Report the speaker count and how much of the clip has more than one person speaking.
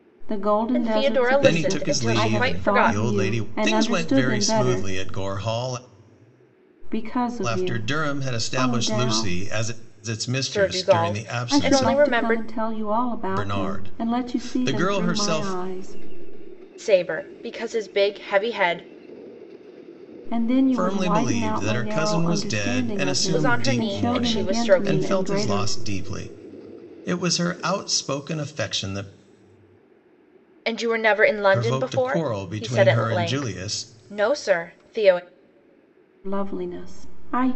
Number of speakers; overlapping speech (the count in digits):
3, about 47%